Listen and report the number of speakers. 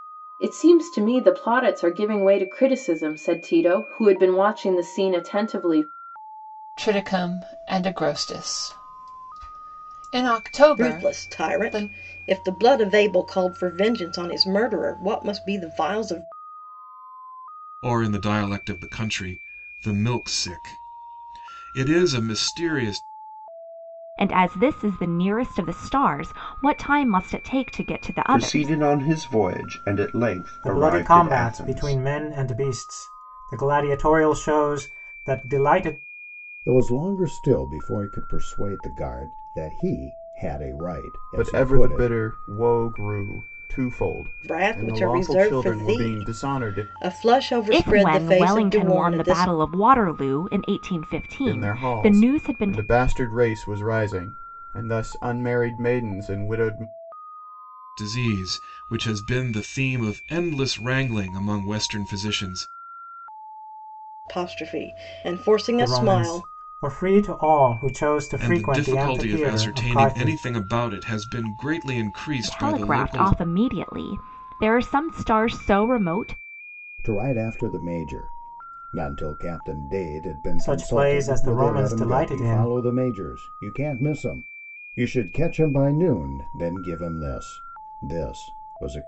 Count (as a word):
nine